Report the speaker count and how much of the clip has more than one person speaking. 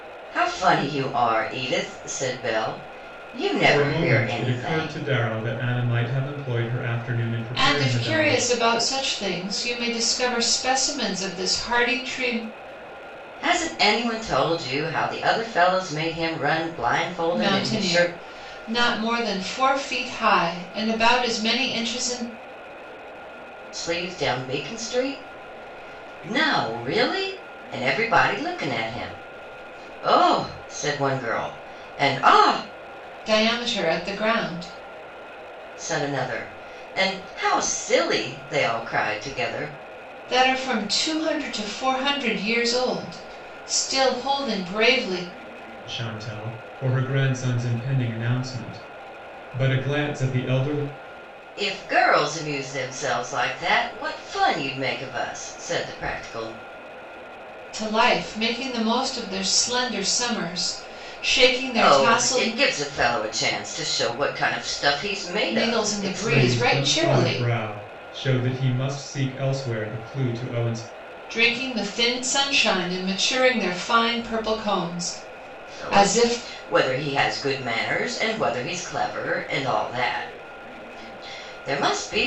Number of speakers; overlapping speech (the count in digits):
3, about 8%